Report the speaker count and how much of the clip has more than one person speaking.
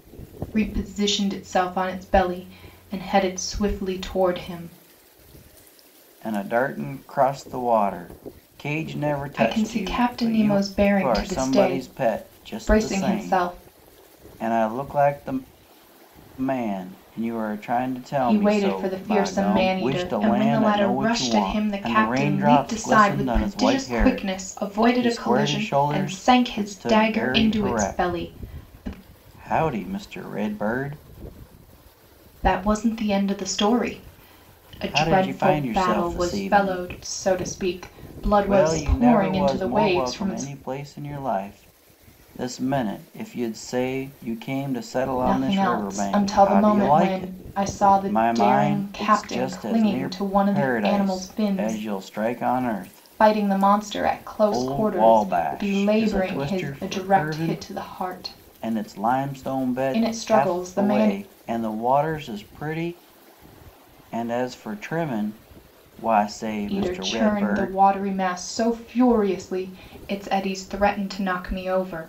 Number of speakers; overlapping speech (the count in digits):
2, about 46%